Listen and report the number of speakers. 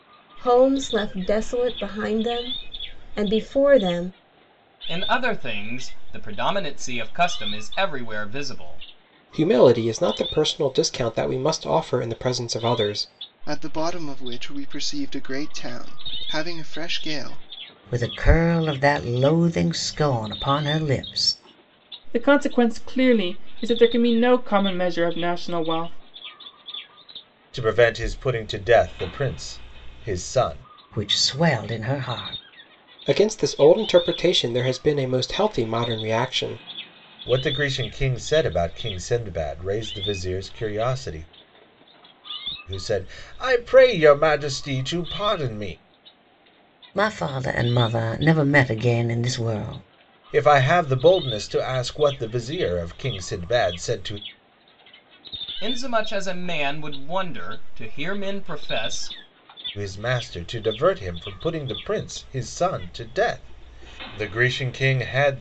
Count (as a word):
seven